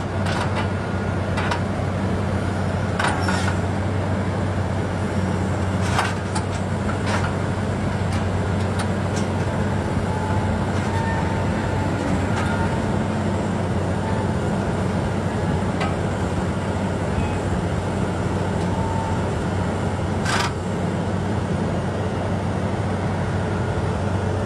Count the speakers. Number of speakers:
0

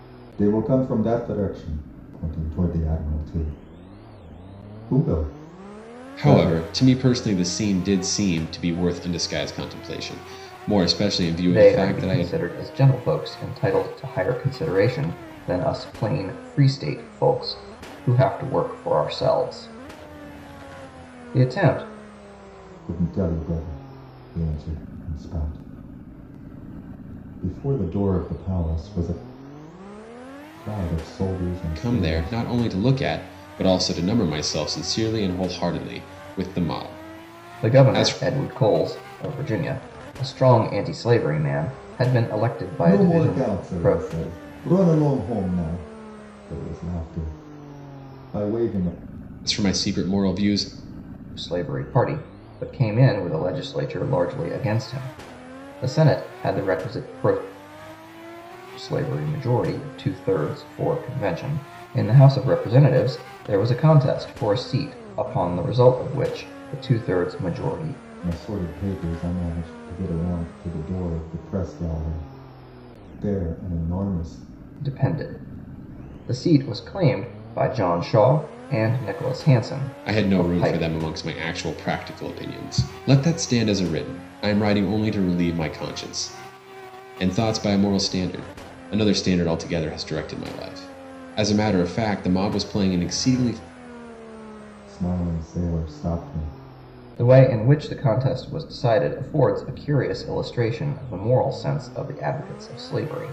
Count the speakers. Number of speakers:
3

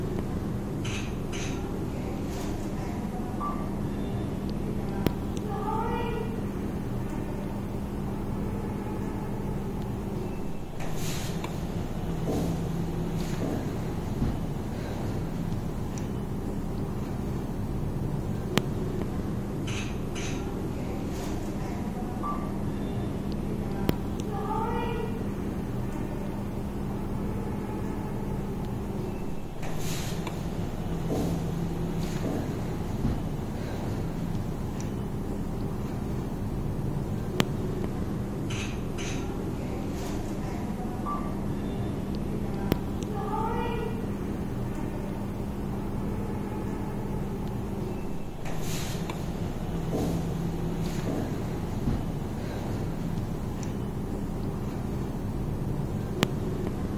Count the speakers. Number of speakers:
0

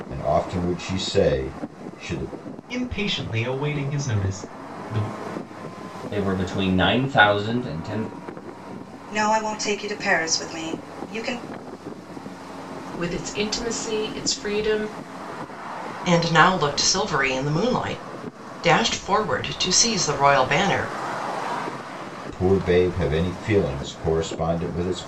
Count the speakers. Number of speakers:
6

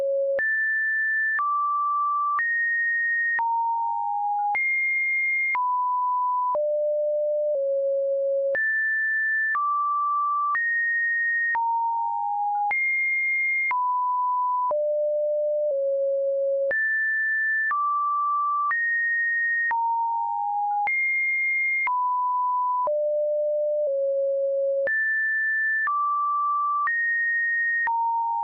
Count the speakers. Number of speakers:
0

